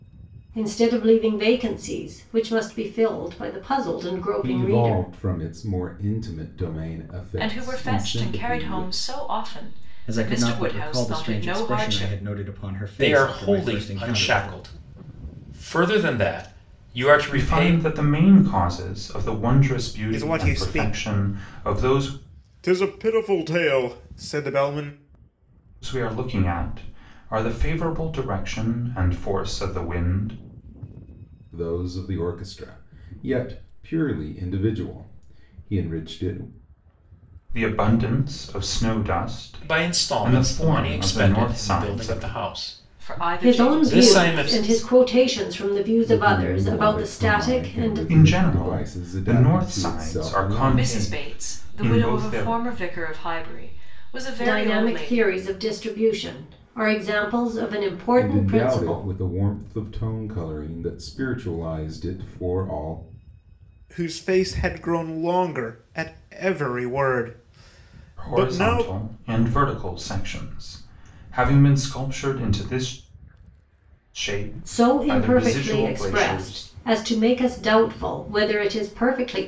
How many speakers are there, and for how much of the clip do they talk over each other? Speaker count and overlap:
seven, about 31%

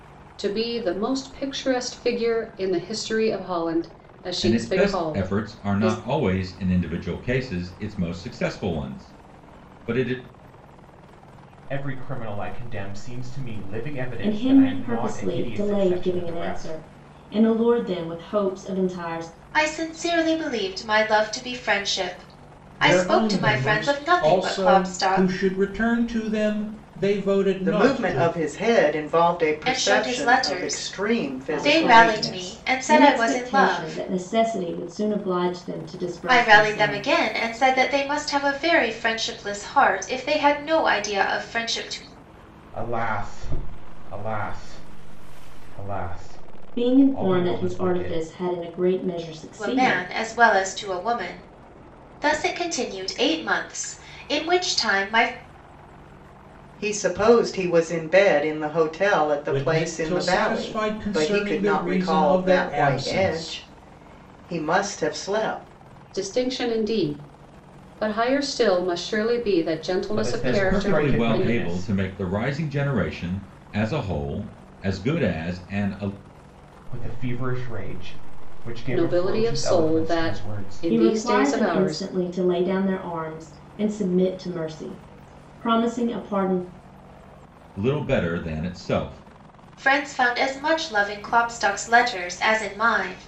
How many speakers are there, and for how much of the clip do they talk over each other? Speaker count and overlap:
seven, about 26%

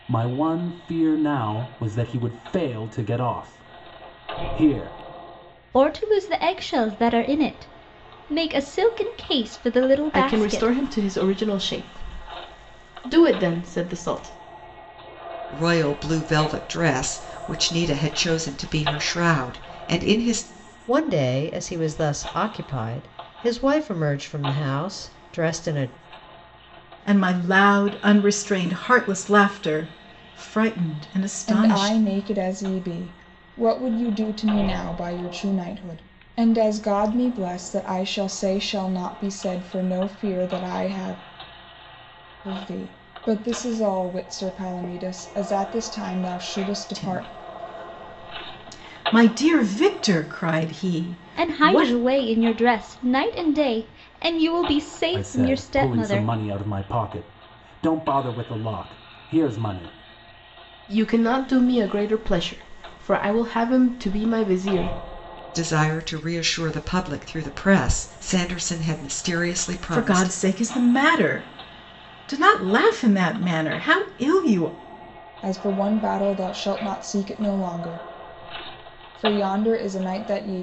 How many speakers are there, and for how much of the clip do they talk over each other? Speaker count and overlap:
seven, about 5%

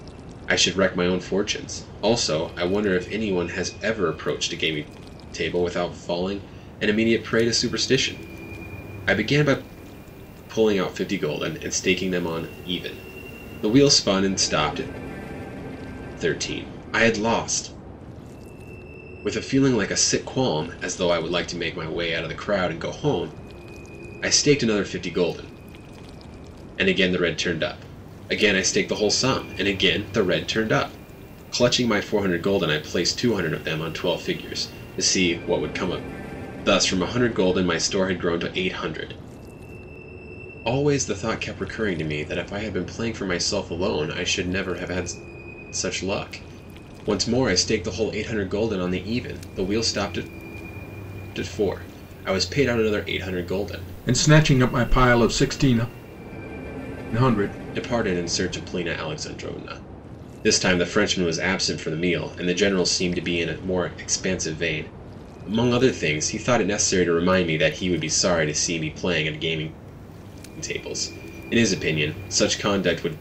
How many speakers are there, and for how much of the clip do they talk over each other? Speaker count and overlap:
one, no overlap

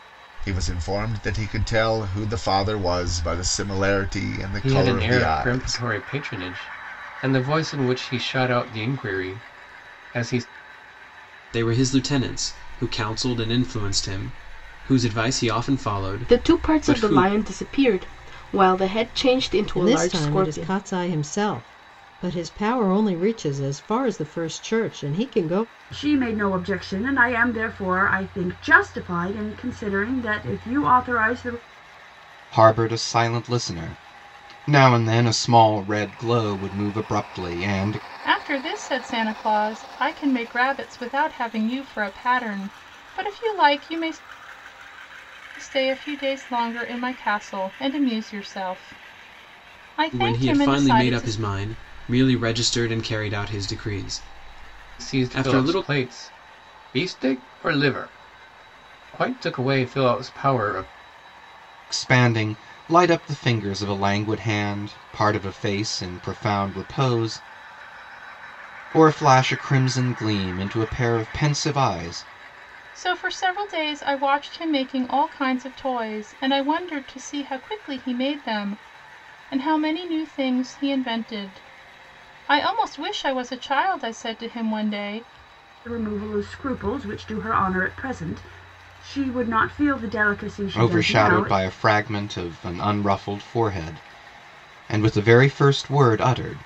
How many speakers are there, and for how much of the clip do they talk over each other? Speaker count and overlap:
eight, about 7%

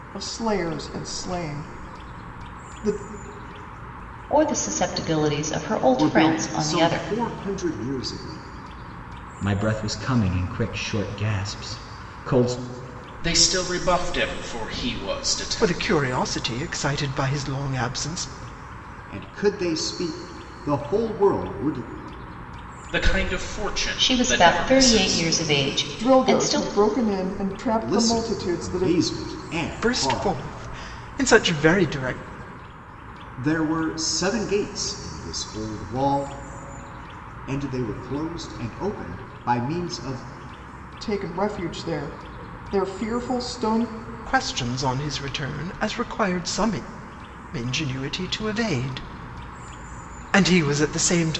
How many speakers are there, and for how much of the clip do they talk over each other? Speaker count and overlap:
six, about 11%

